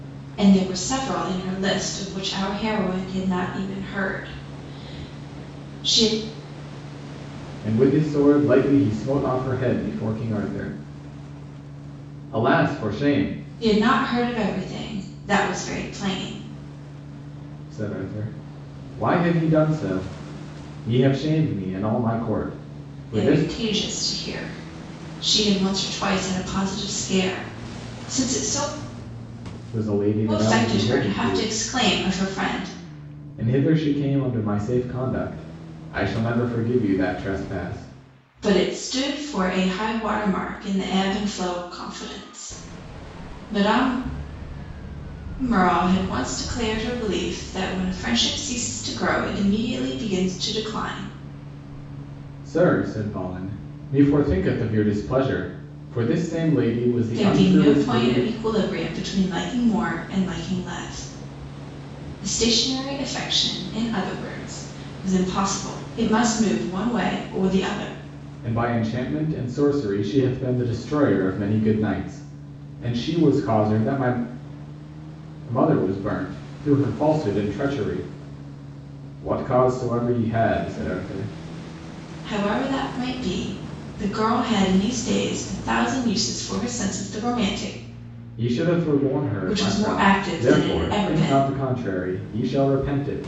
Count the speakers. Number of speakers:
two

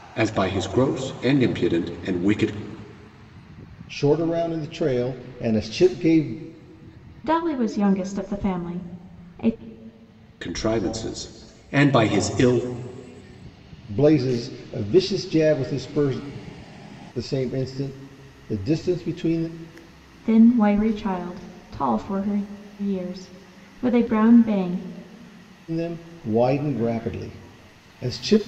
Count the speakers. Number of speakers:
three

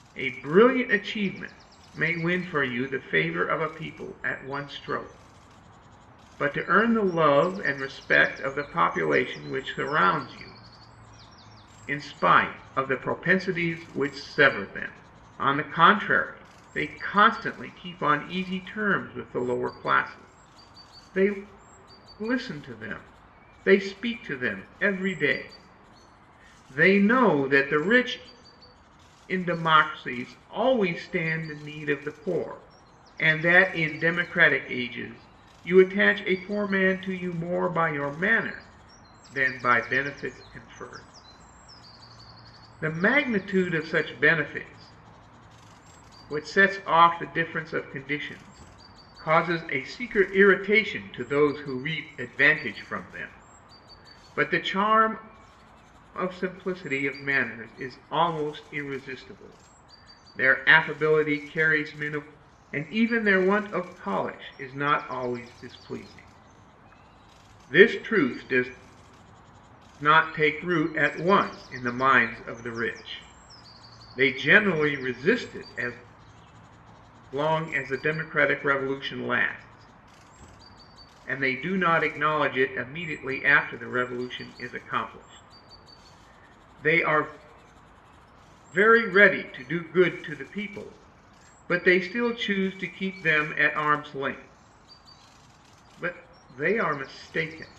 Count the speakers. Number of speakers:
one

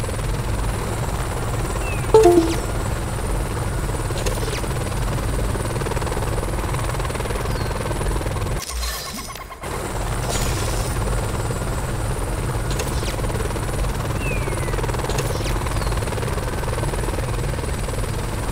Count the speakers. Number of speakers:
zero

